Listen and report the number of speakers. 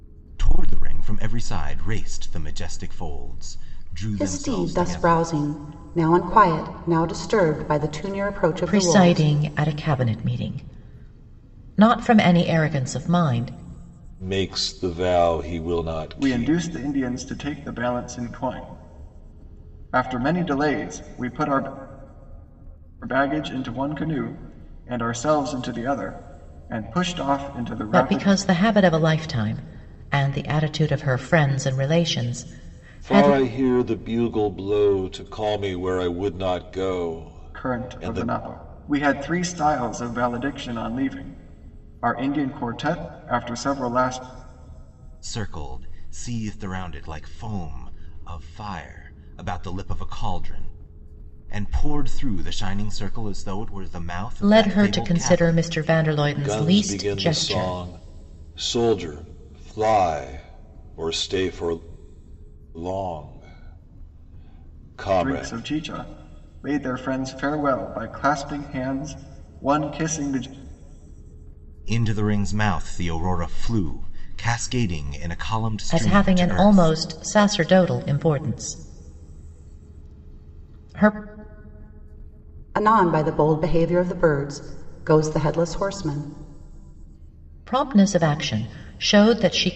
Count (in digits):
5